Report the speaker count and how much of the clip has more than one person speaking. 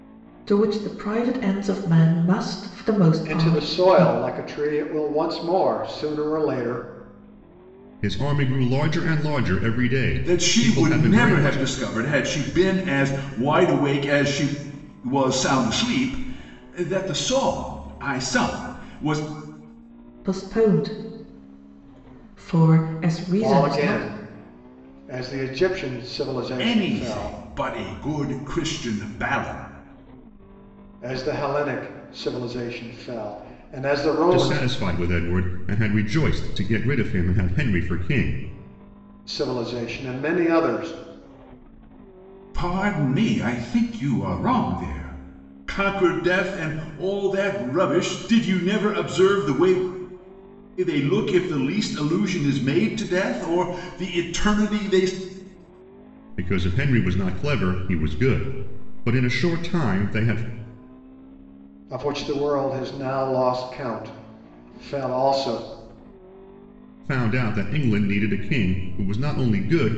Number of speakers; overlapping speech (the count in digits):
4, about 6%